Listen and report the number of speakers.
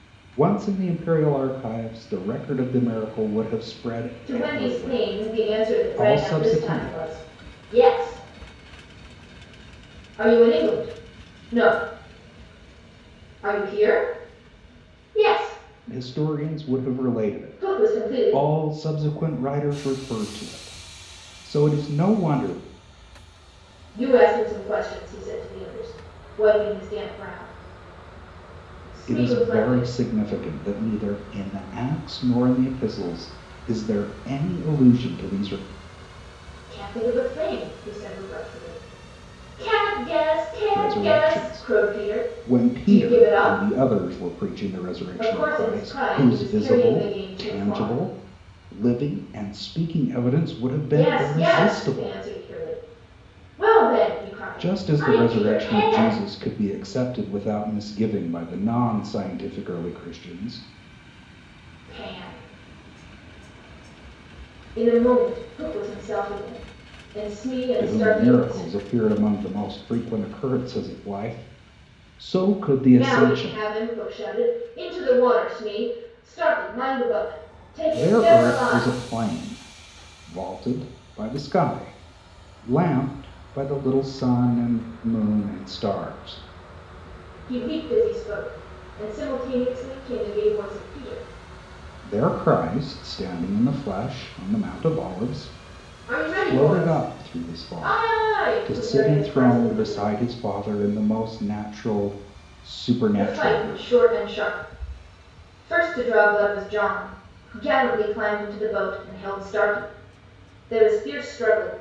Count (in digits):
2